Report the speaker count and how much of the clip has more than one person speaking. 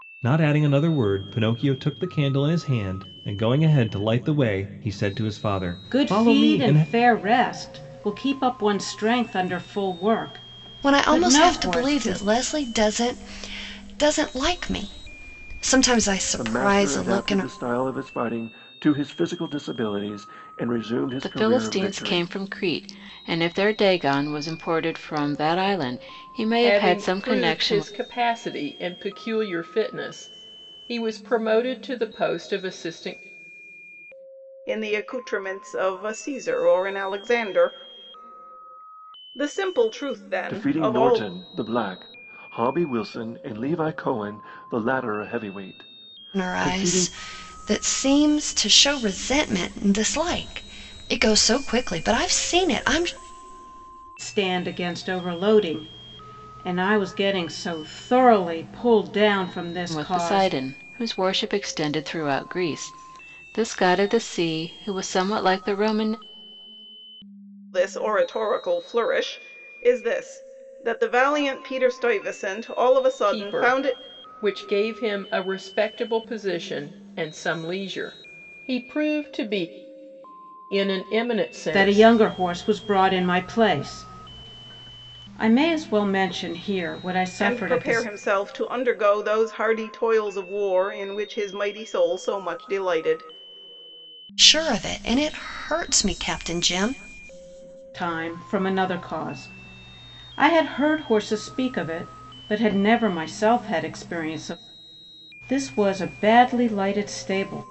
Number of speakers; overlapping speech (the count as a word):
seven, about 10%